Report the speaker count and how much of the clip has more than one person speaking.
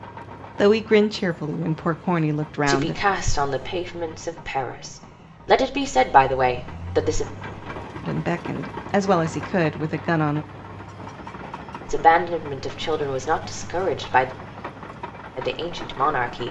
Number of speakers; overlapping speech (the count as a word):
two, about 2%